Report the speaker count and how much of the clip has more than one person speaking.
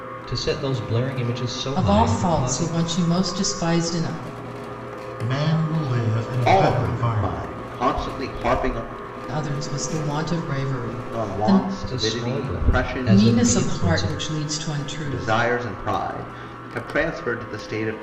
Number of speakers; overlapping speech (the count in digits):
4, about 29%